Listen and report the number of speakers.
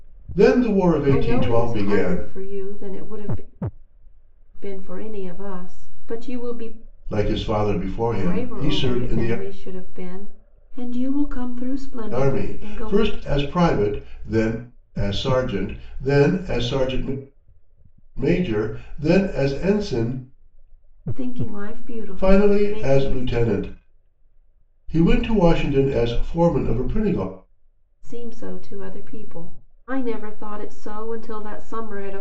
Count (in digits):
2